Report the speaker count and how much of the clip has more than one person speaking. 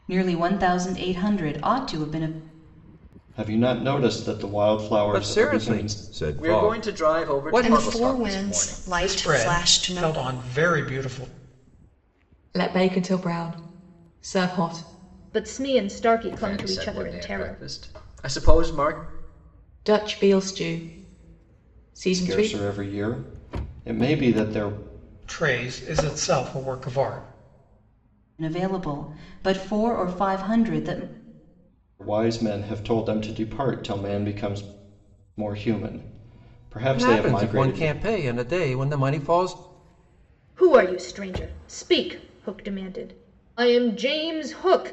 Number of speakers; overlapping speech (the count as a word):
eight, about 17%